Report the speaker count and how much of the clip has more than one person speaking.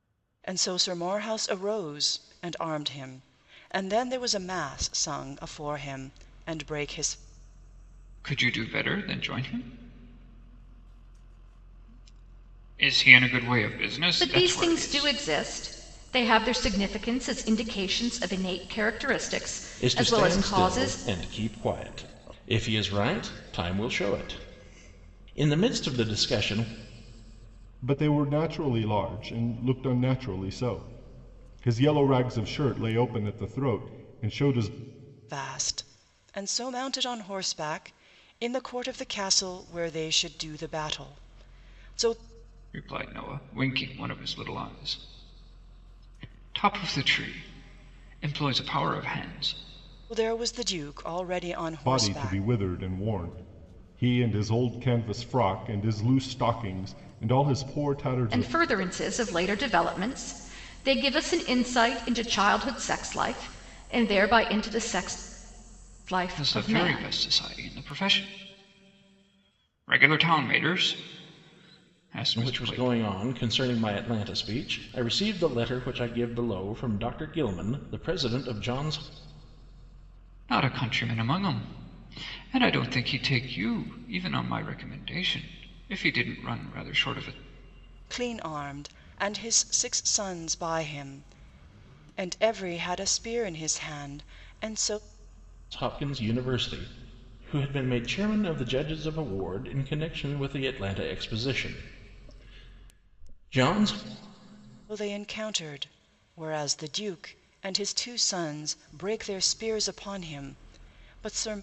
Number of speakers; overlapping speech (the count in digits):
5, about 4%